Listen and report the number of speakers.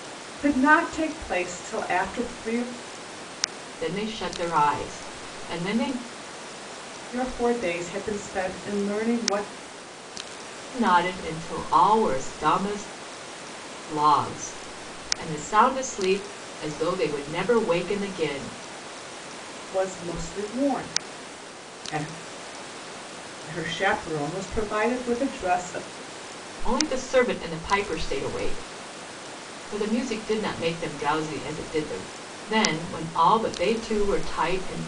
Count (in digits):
2